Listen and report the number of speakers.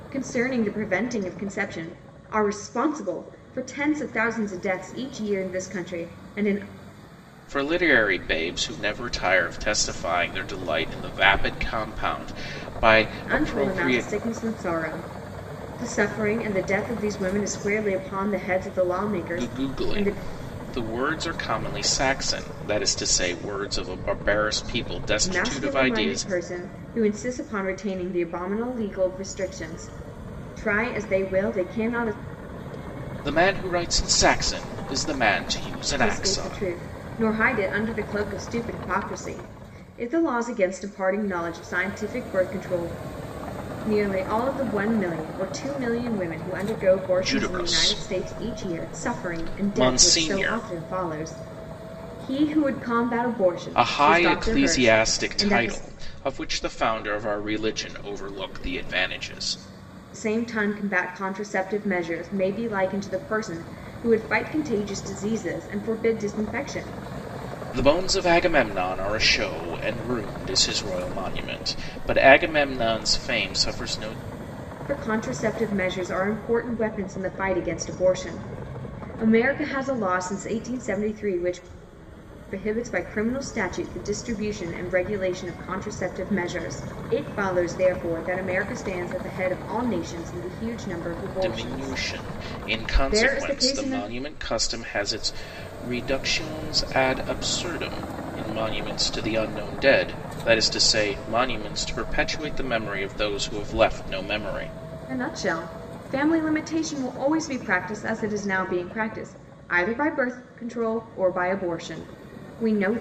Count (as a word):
two